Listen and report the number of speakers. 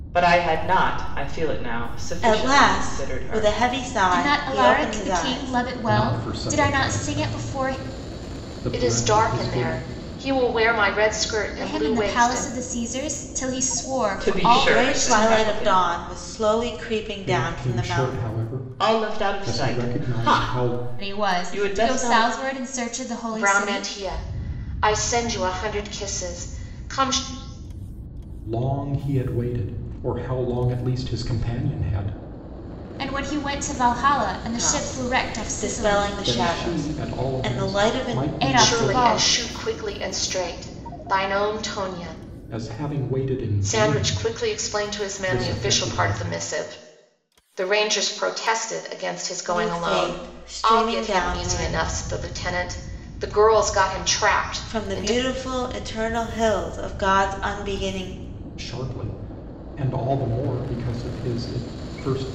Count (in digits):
5